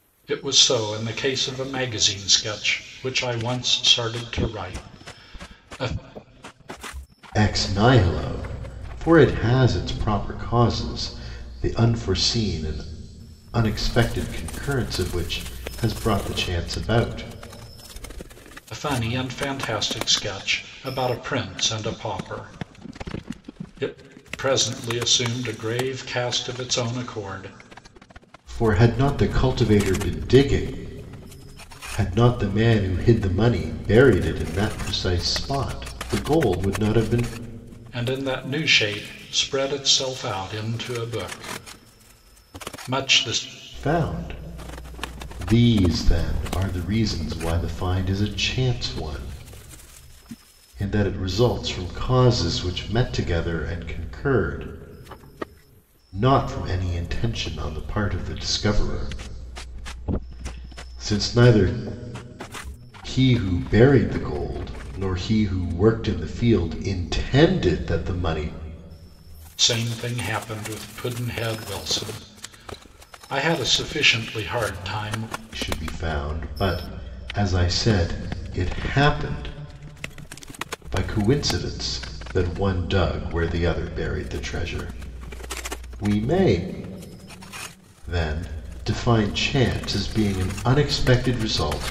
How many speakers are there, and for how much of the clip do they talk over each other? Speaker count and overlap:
2, no overlap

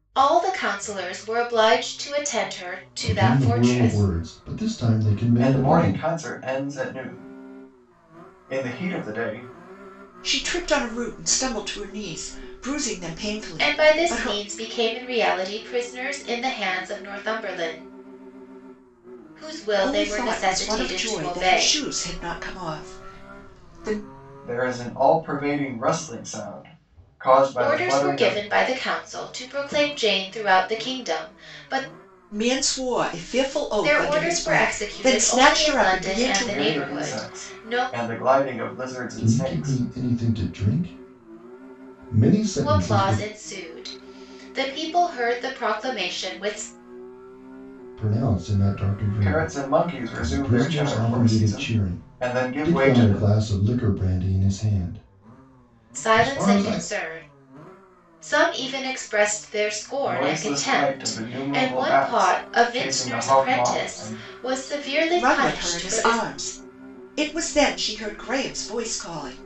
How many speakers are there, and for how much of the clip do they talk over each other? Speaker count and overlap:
4, about 30%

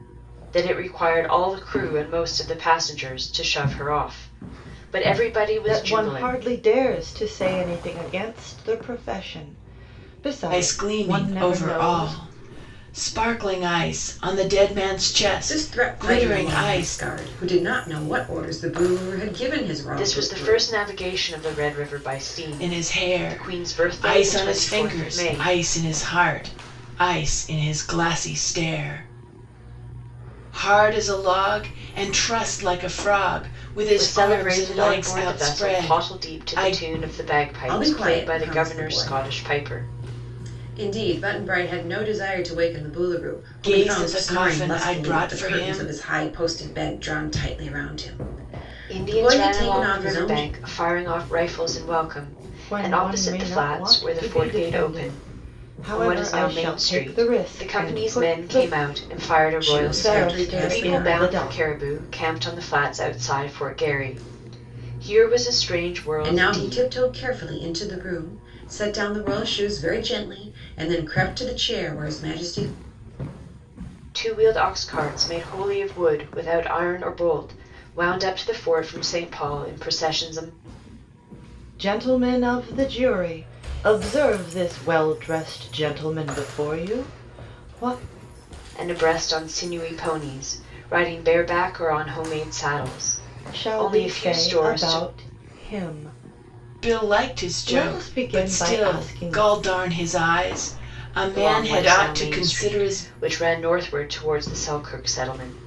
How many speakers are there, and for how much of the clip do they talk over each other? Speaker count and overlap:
4, about 30%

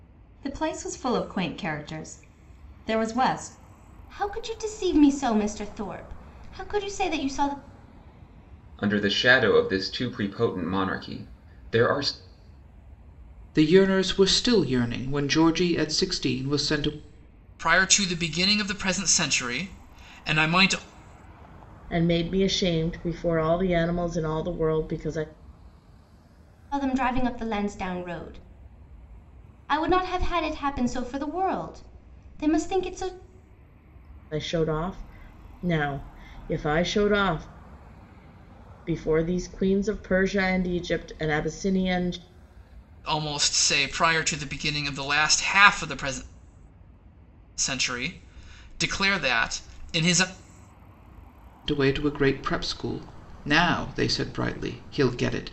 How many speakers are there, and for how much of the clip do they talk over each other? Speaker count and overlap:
6, no overlap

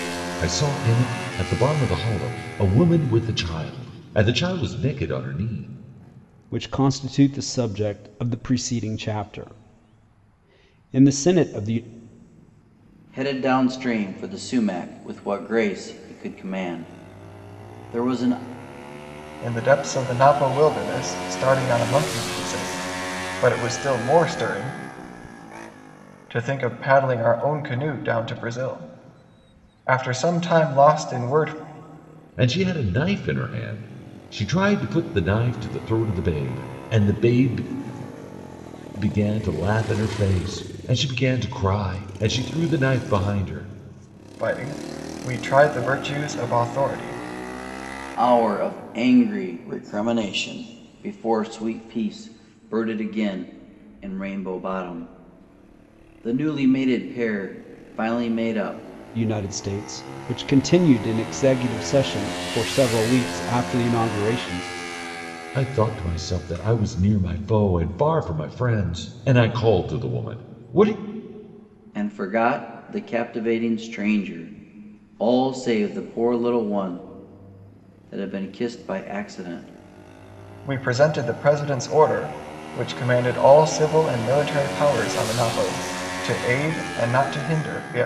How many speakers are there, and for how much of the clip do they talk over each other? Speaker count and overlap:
4, no overlap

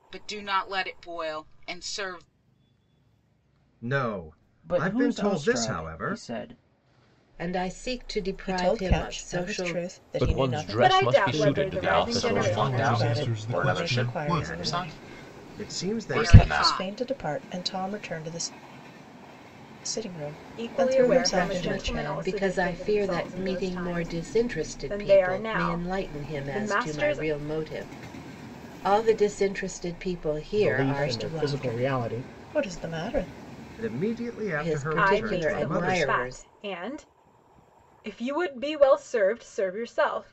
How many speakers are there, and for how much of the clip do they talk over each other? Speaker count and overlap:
10, about 49%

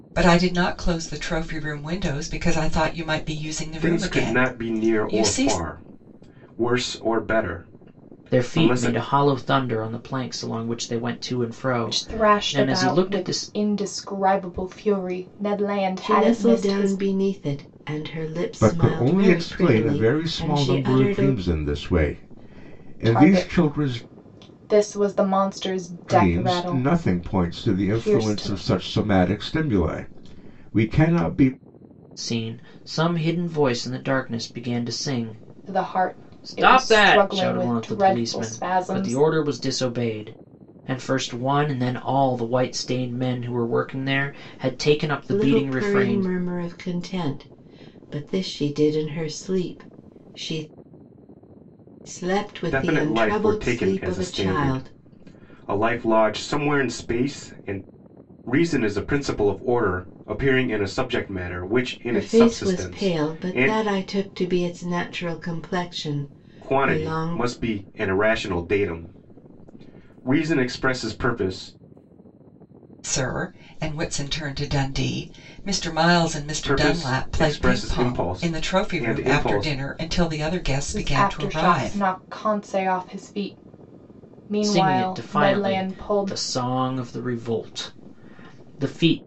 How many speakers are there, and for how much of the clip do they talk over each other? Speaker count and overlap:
6, about 31%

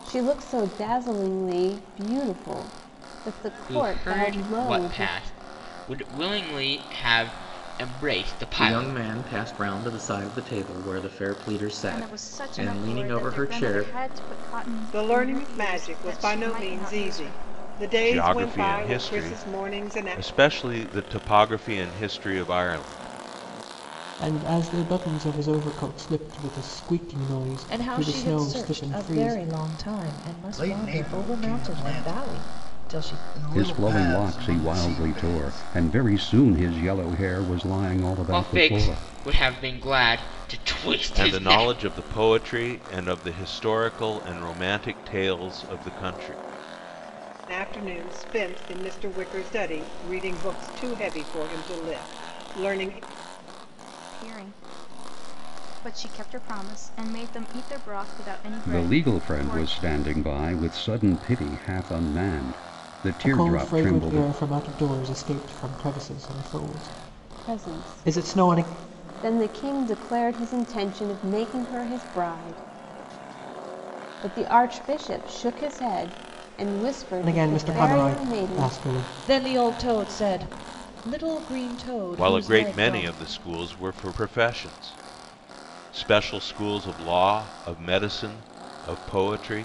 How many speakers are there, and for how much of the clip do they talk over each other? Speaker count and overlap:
10, about 26%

